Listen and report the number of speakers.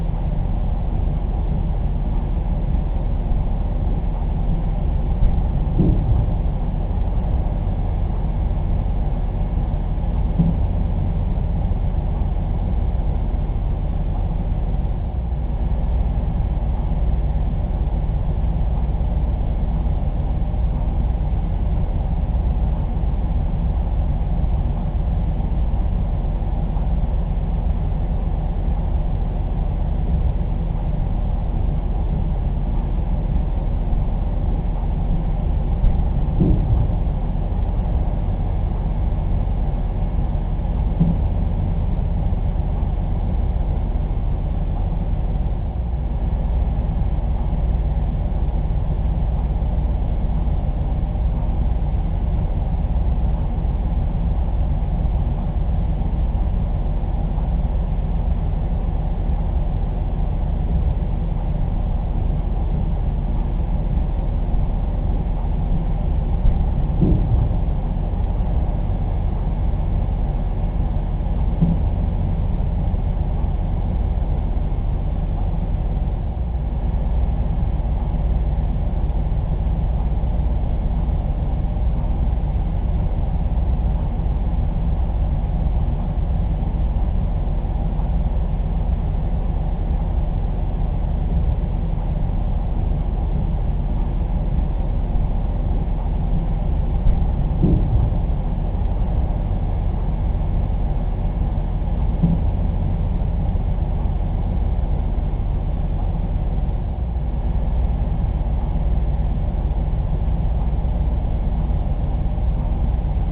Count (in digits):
0